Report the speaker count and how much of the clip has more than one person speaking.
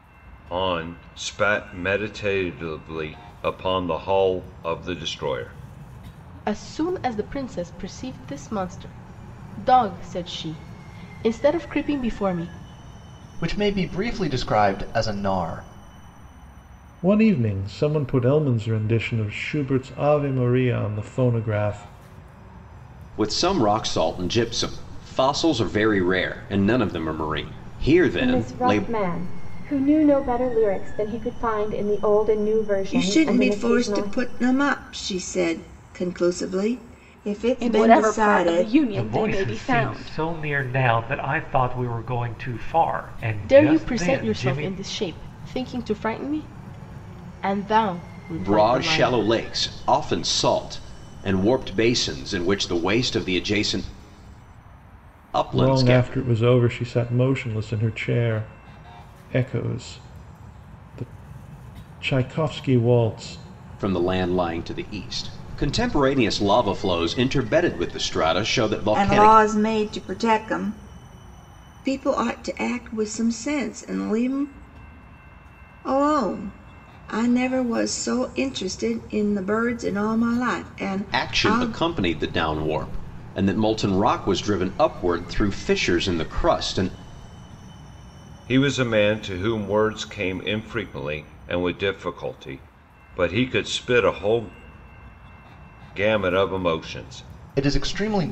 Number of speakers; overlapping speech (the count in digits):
9, about 9%